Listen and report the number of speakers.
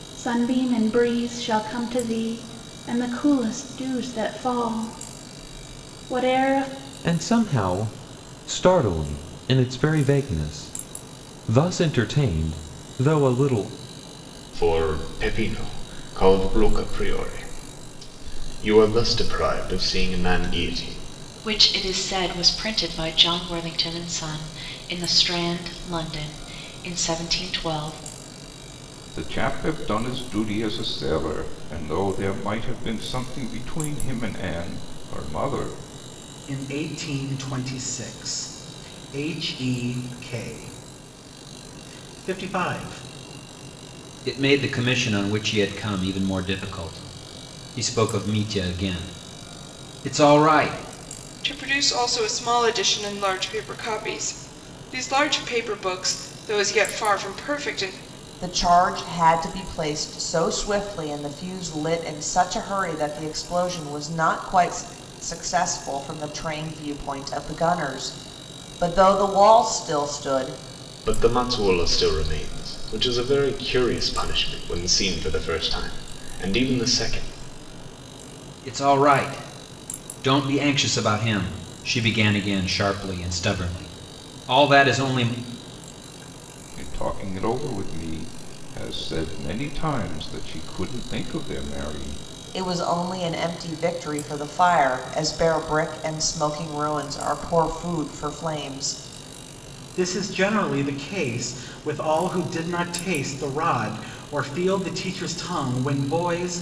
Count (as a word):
nine